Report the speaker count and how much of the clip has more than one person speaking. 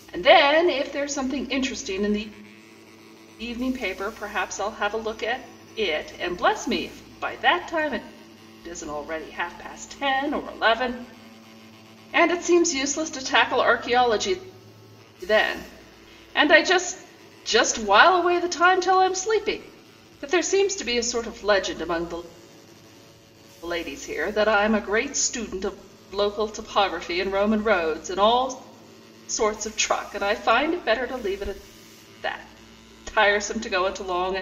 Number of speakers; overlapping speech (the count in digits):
1, no overlap